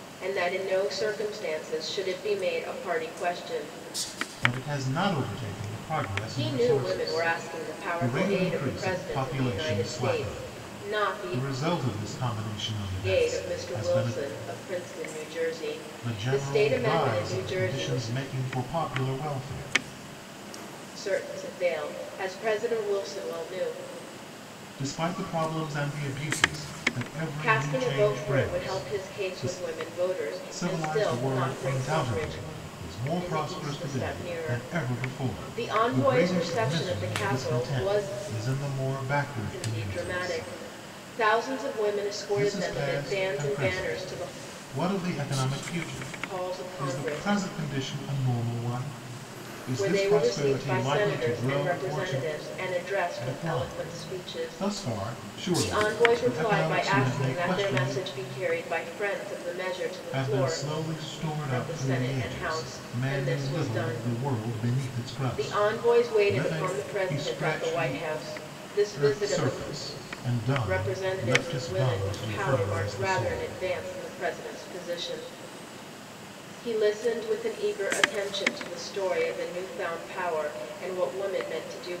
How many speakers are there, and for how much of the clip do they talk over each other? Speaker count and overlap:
2, about 45%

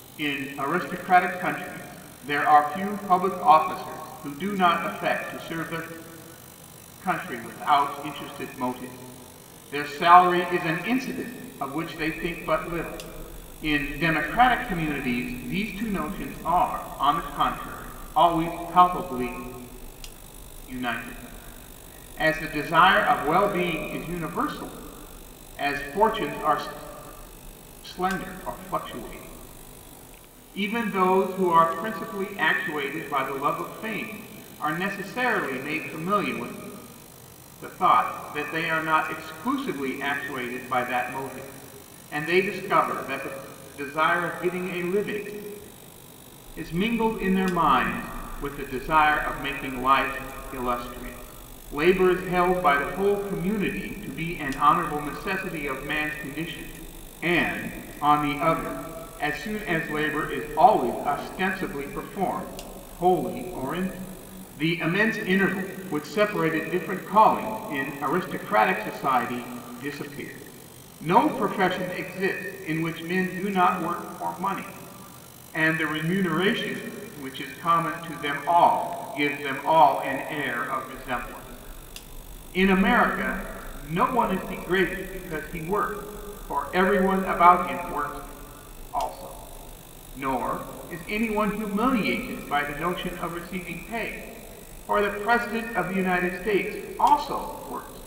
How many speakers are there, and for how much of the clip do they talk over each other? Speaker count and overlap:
1, no overlap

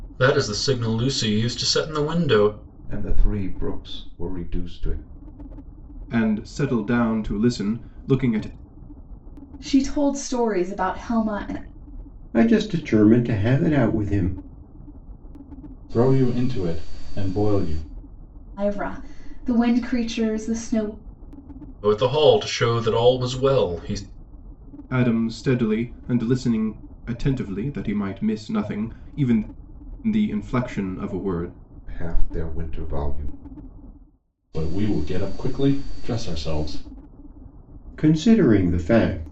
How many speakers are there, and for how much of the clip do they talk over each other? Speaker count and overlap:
6, no overlap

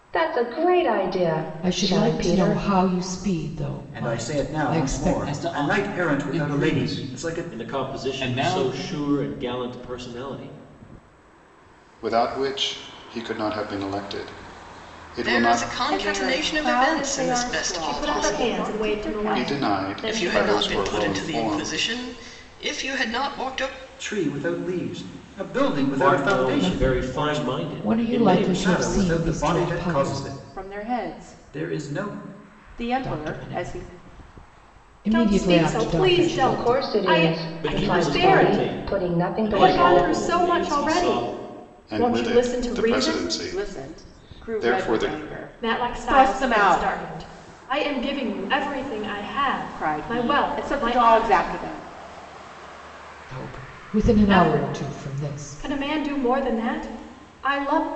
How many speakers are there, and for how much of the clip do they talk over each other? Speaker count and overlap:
9, about 57%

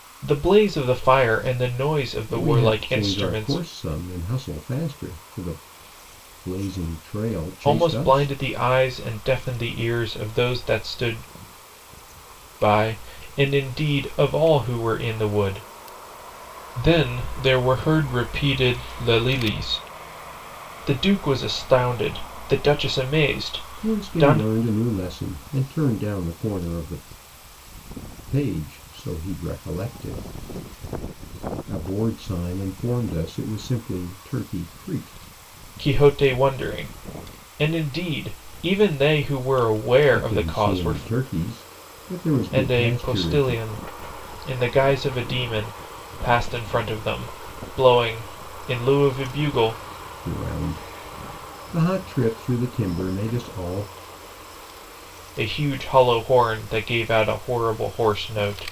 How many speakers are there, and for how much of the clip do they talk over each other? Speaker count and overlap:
2, about 8%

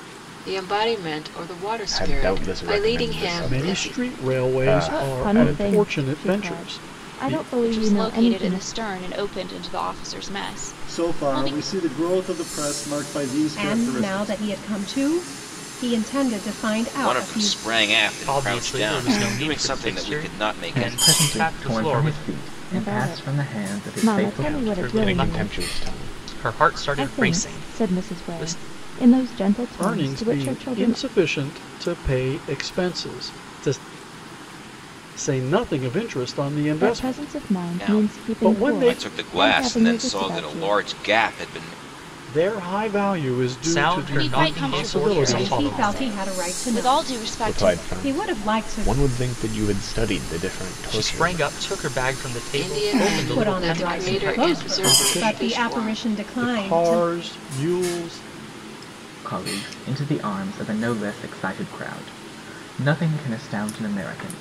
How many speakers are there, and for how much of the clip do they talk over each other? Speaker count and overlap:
10, about 52%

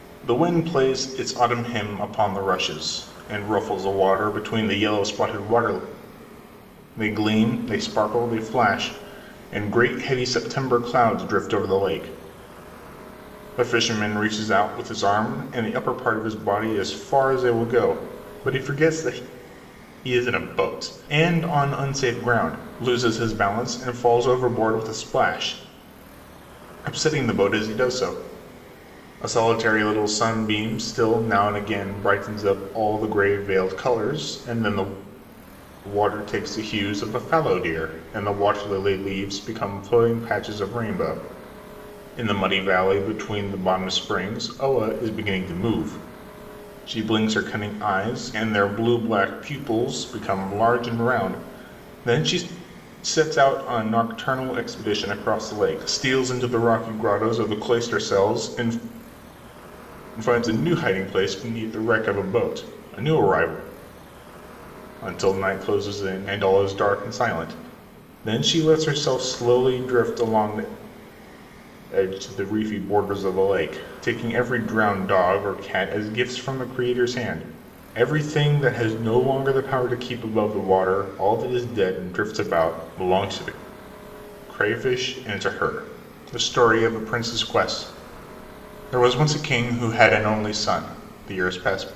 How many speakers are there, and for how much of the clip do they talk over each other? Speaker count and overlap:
1, no overlap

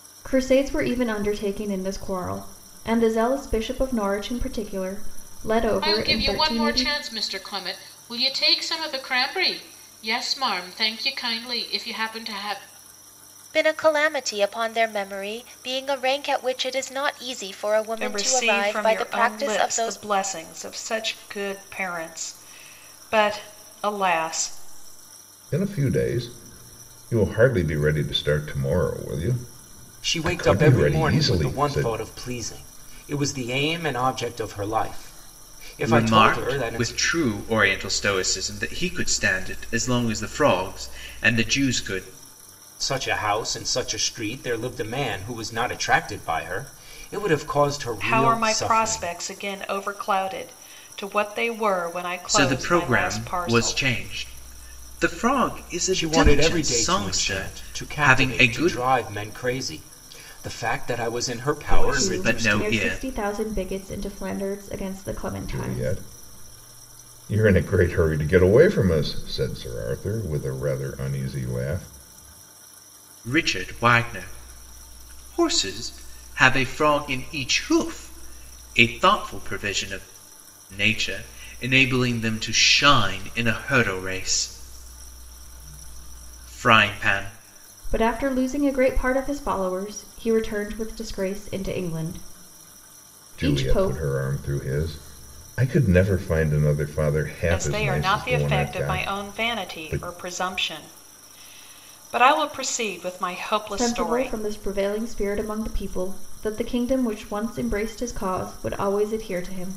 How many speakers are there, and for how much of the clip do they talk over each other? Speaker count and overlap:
7, about 16%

